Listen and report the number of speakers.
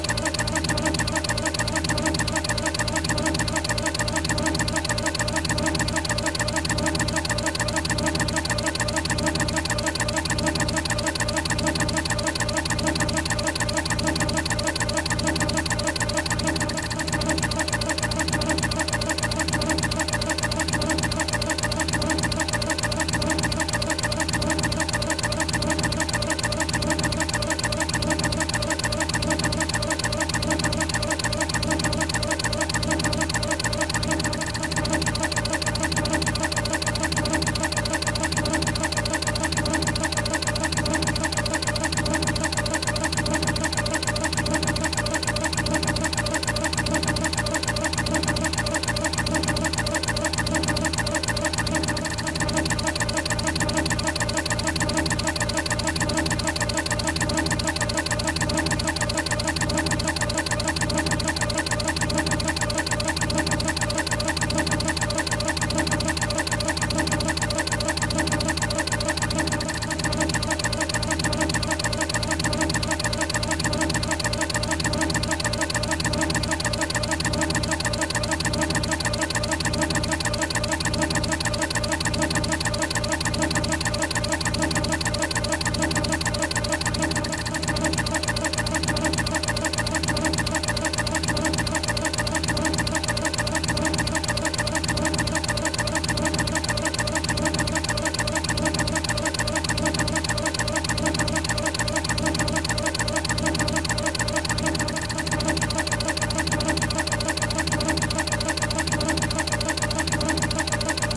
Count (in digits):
0